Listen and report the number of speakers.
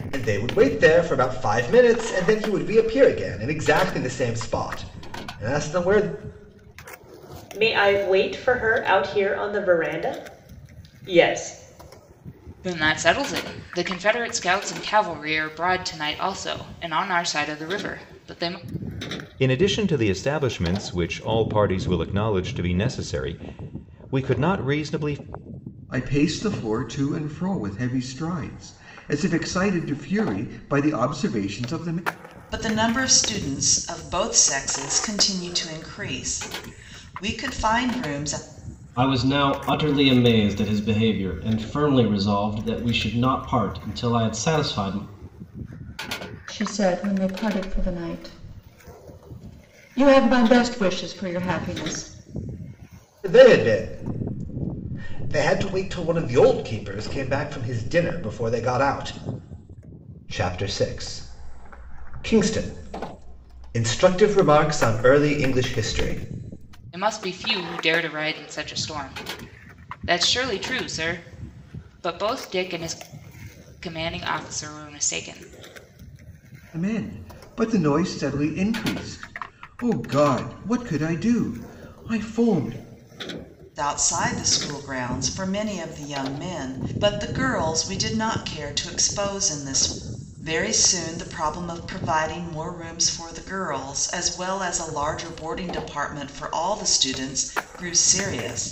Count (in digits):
8